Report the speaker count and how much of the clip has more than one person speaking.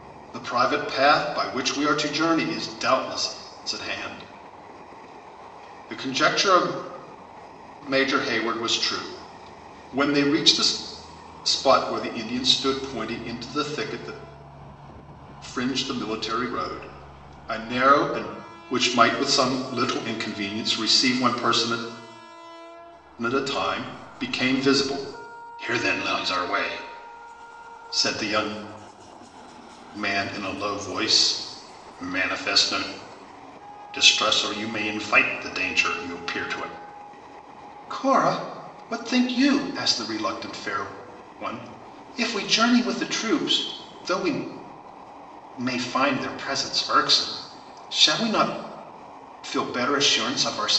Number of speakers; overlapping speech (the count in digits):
1, no overlap